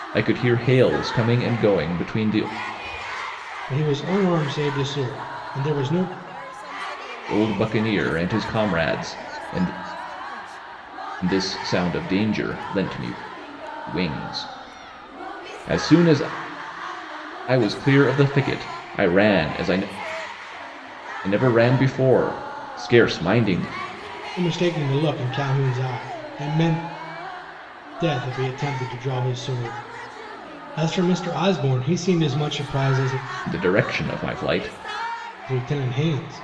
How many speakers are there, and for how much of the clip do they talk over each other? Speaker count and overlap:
2, no overlap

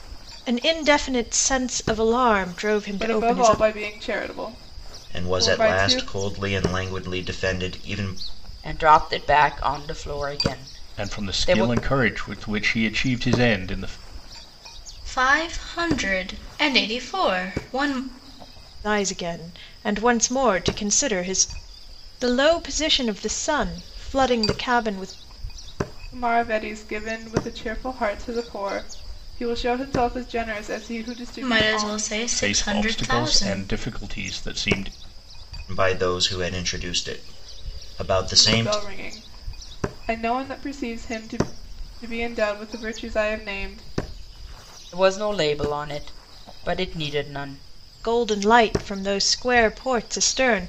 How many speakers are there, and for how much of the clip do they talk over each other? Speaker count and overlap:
6, about 10%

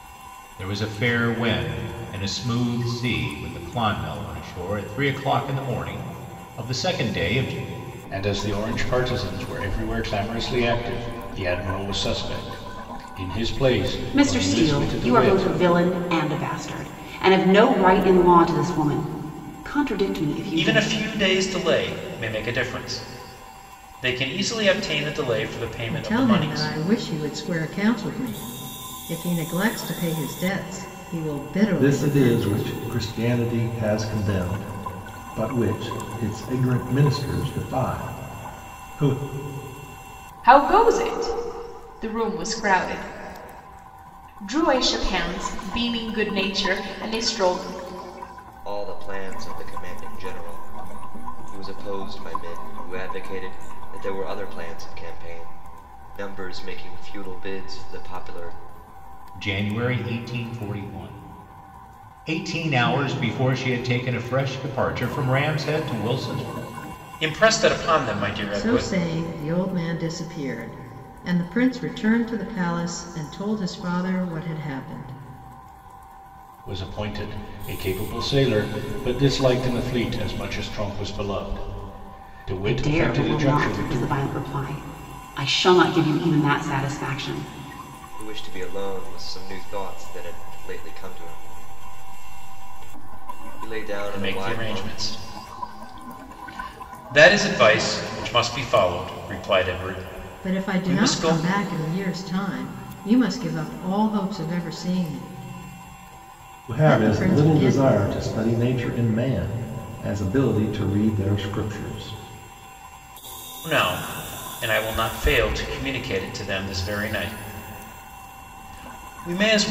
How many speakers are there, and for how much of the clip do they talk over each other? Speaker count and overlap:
8, about 7%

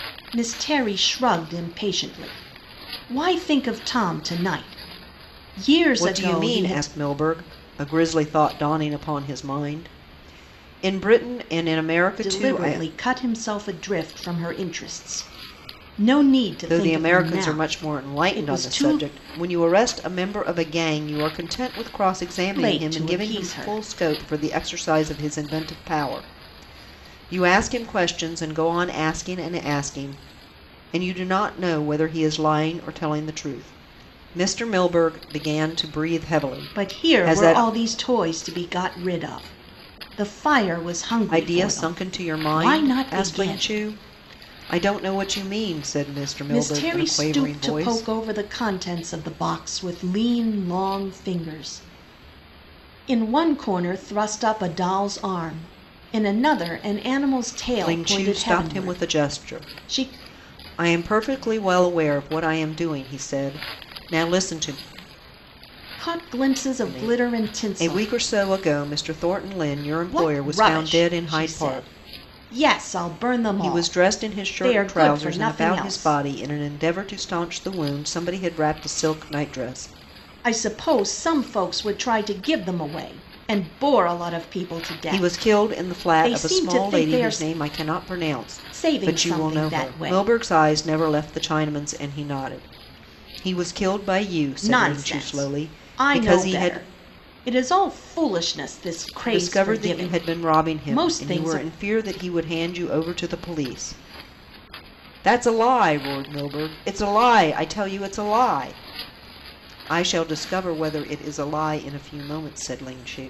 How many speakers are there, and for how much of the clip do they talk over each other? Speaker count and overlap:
2, about 24%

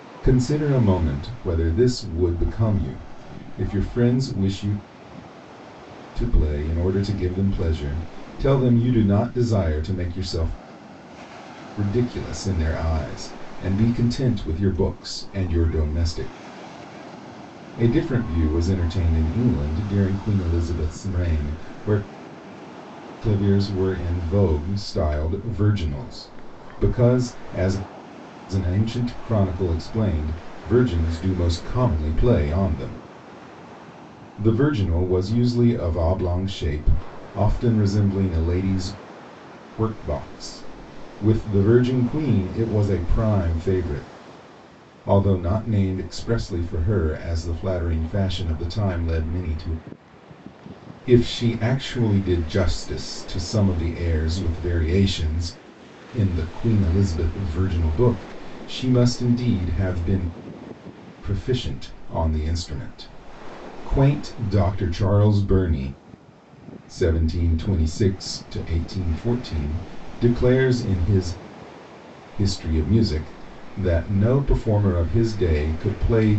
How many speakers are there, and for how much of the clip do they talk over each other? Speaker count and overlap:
1, no overlap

